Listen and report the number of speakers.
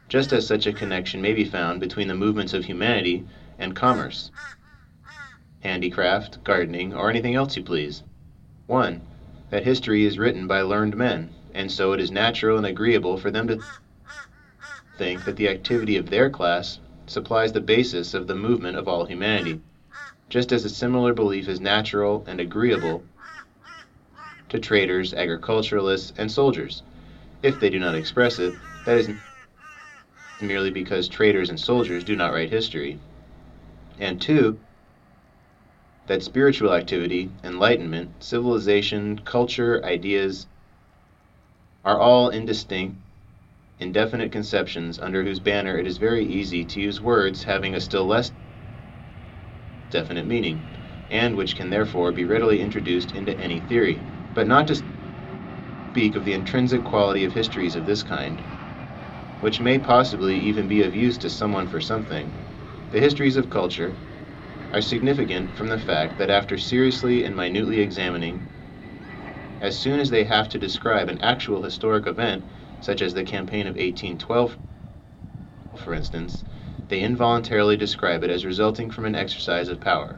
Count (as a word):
one